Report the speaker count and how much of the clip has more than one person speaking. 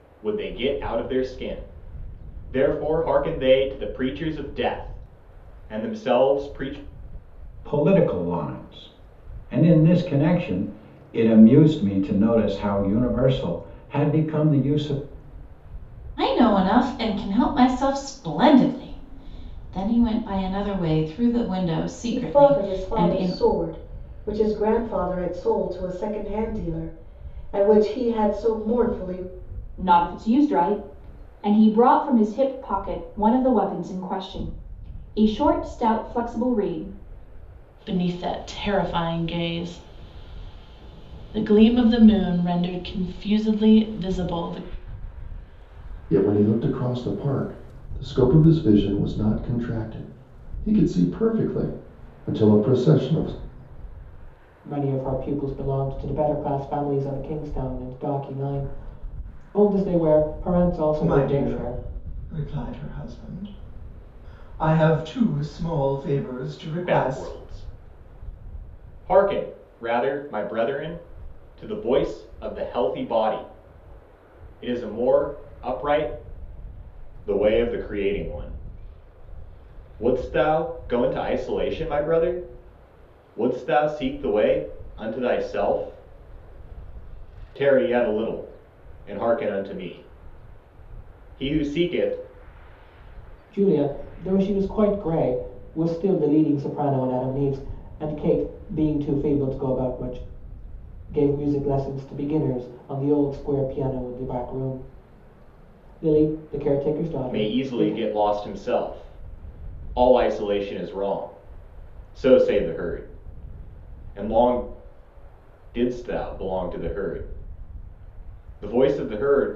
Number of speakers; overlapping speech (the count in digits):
9, about 3%